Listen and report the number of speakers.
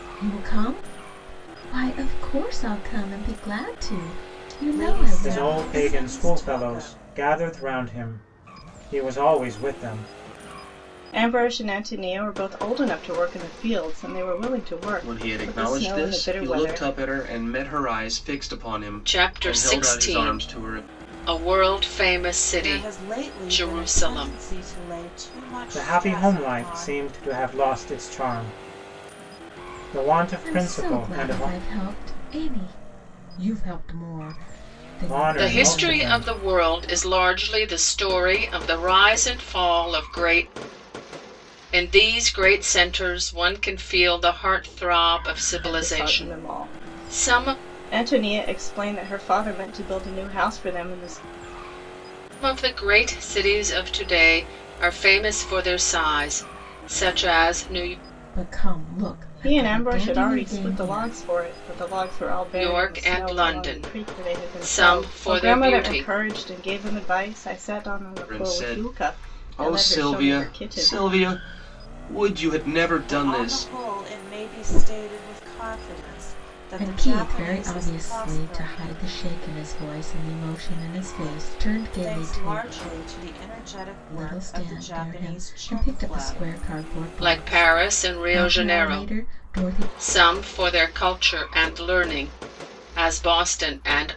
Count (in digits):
6